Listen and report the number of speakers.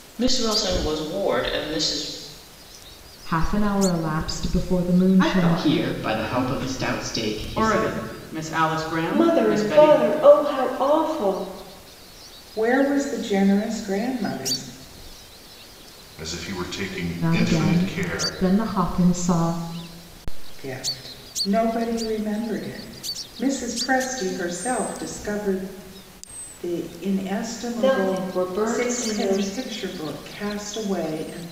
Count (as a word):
eight